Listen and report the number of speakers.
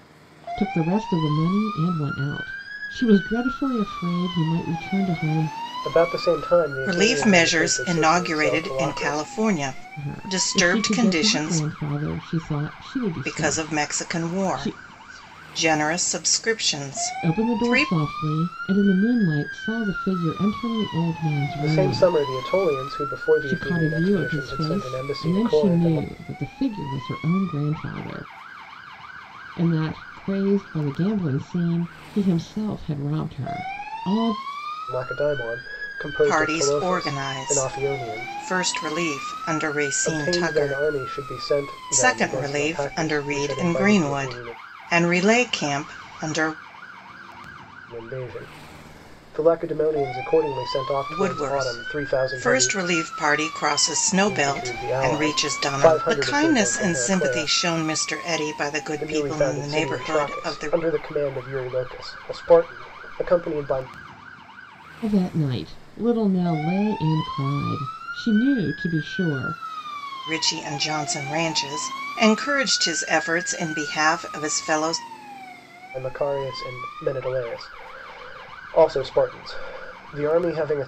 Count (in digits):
3